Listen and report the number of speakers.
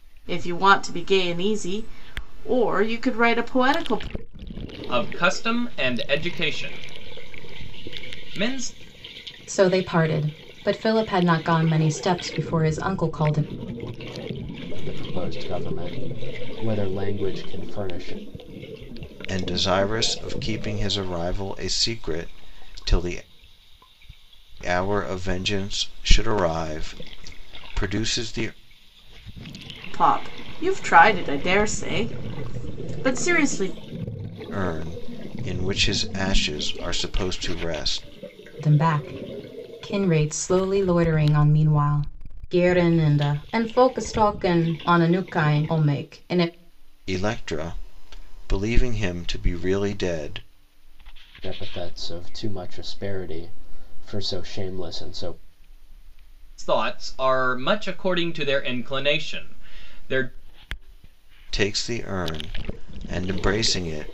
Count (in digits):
5